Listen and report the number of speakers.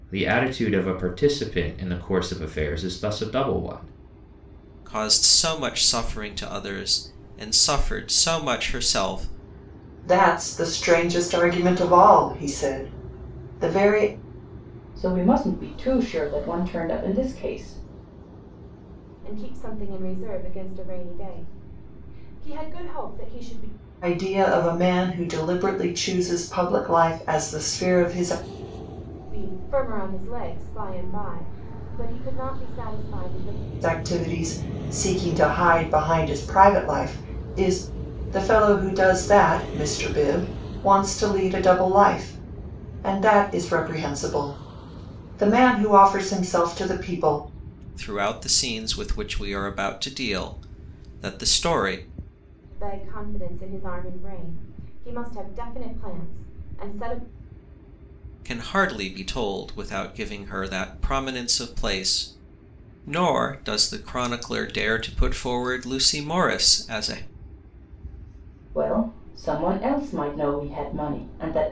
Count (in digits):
5